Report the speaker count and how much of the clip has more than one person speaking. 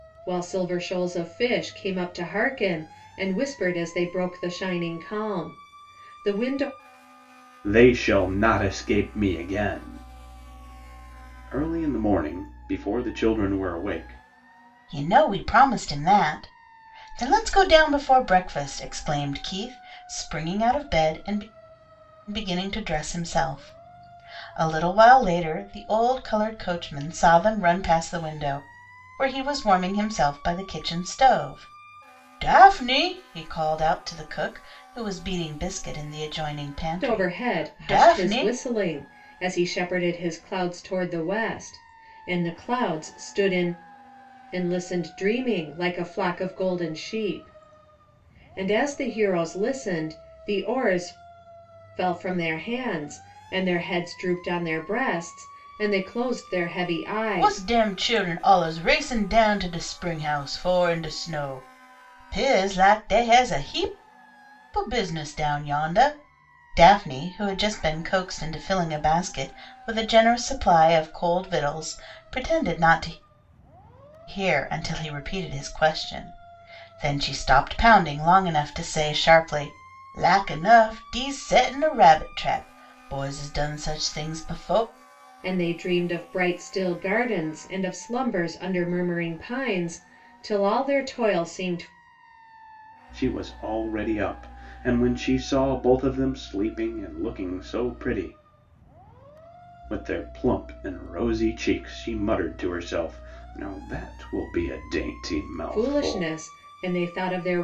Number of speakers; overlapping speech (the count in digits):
3, about 2%